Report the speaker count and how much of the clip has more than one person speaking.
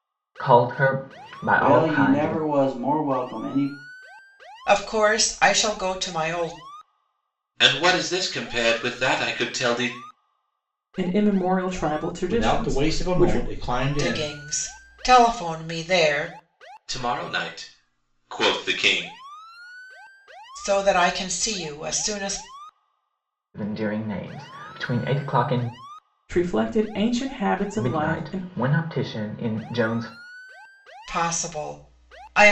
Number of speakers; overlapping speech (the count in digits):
6, about 10%